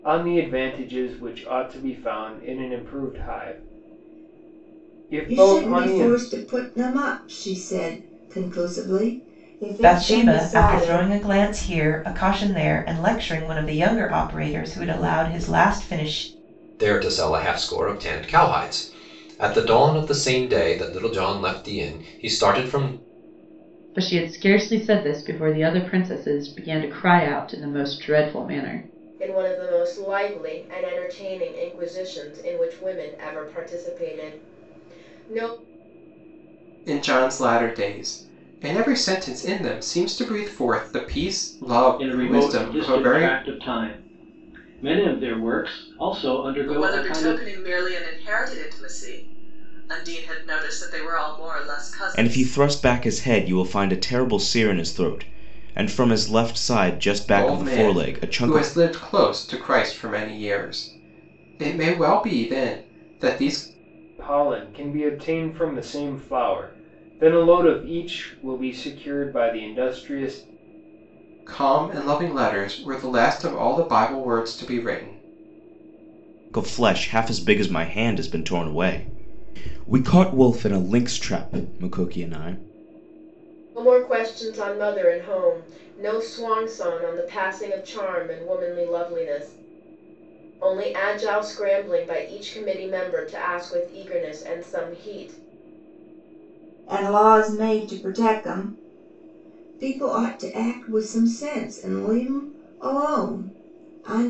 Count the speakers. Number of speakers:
10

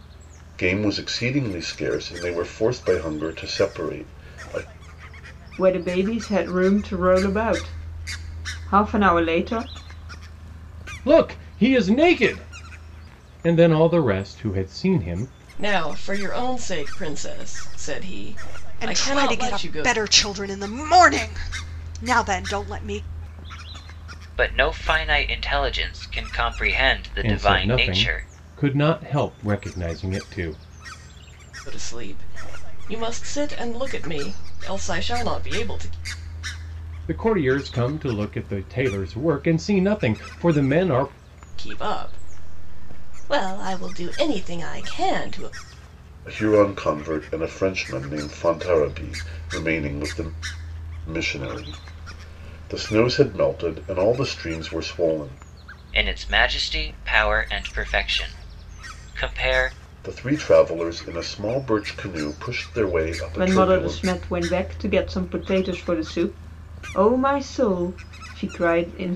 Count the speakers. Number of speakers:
6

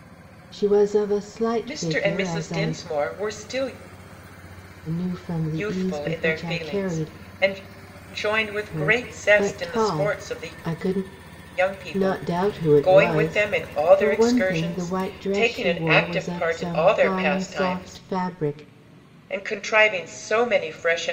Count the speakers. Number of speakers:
2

